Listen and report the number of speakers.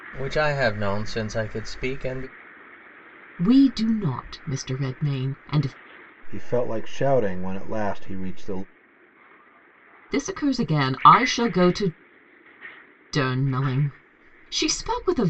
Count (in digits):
3